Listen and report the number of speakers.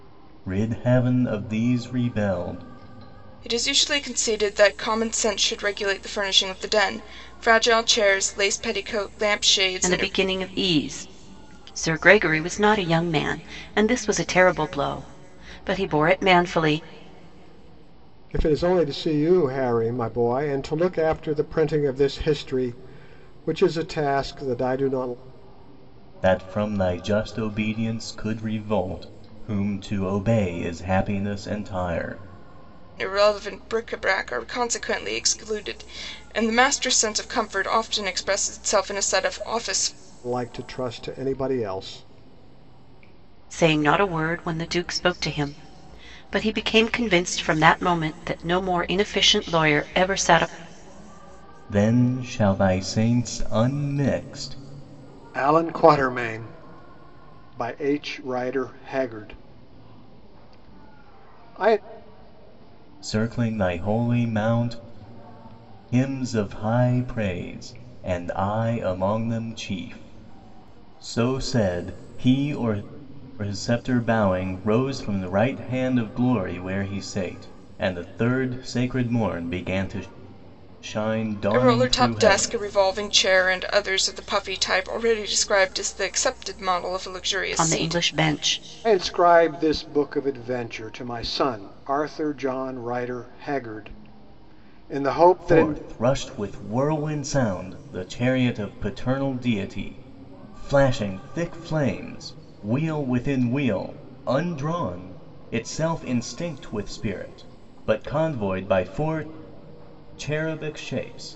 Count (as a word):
four